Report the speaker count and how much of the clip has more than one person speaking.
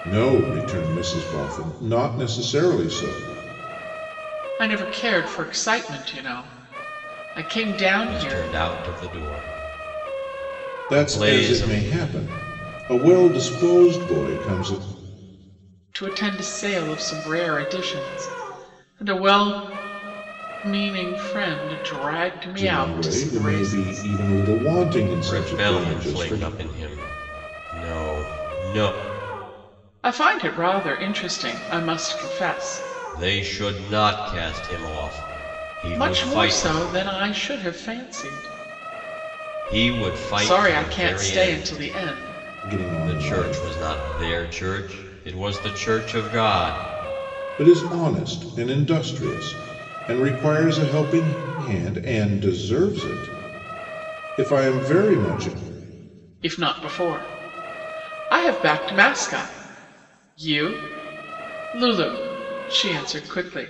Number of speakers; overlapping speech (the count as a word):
three, about 12%